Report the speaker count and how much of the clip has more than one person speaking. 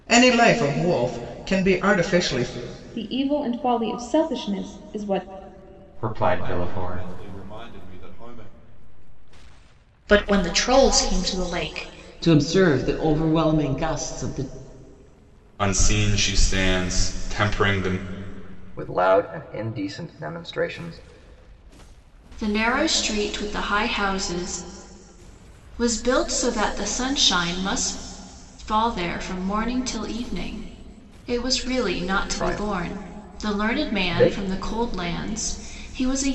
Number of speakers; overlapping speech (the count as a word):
nine, about 8%